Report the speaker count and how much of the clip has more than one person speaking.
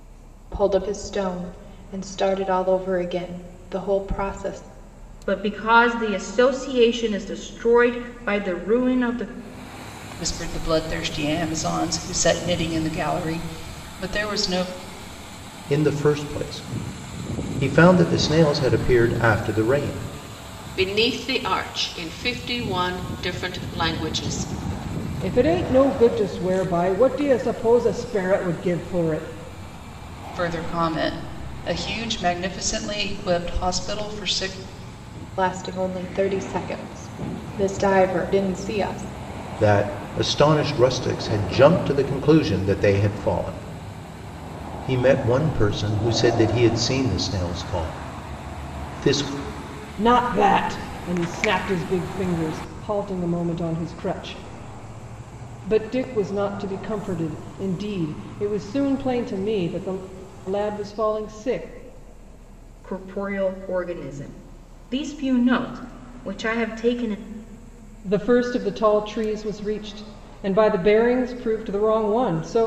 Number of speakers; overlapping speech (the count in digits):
6, no overlap